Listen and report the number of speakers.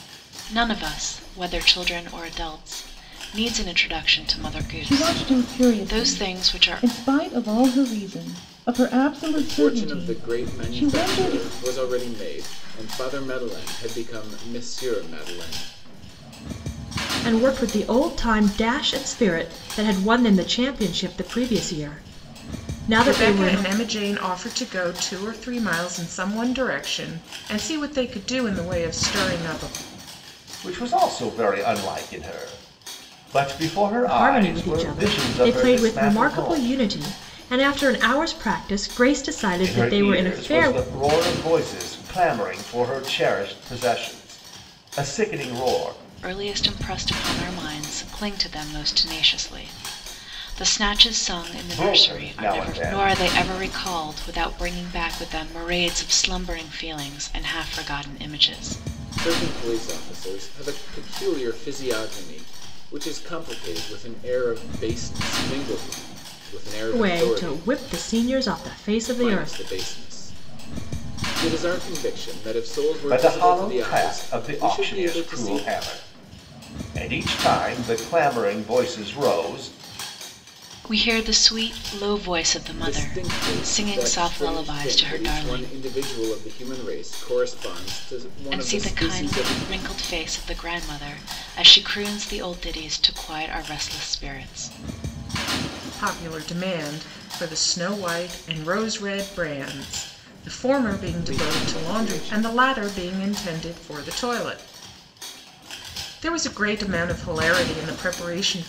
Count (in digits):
6